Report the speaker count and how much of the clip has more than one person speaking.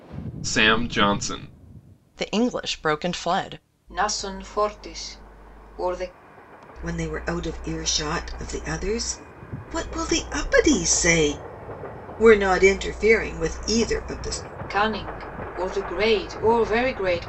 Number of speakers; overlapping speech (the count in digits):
4, no overlap